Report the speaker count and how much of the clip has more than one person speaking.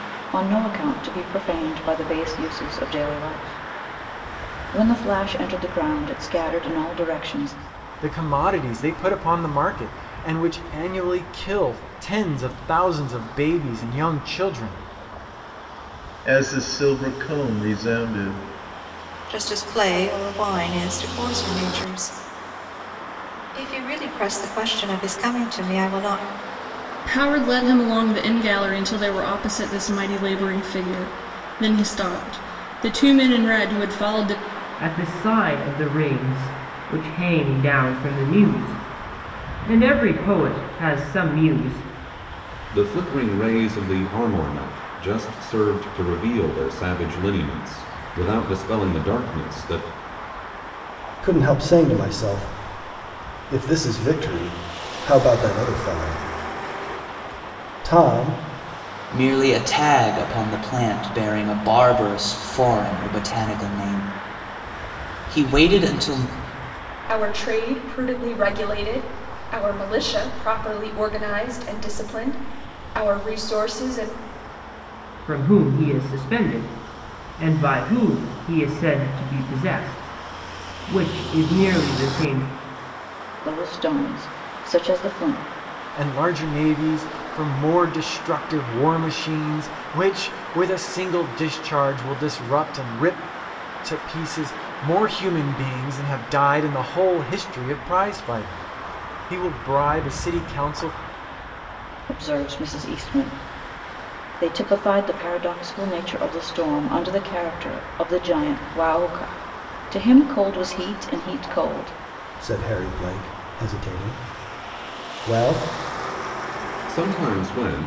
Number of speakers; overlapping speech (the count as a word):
ten, no overlap